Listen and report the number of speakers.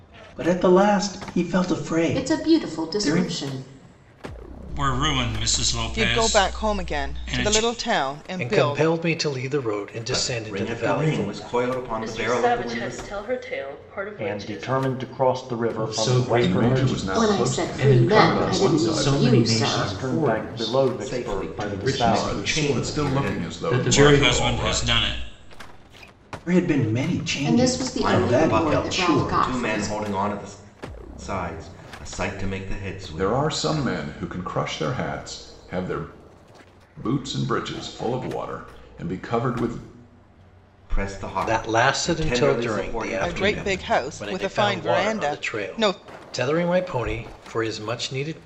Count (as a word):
ten